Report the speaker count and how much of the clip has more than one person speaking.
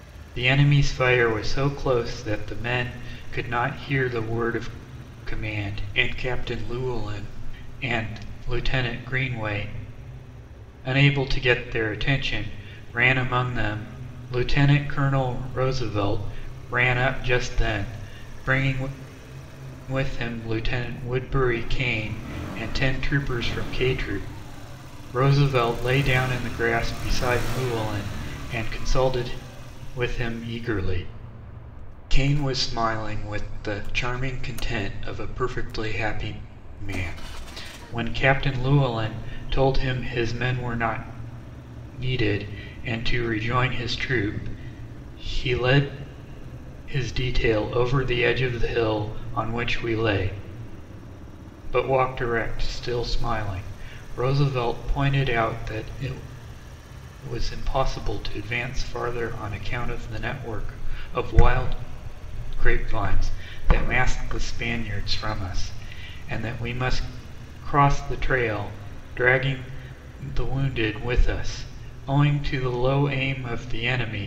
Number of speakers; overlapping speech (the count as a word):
one, no overlap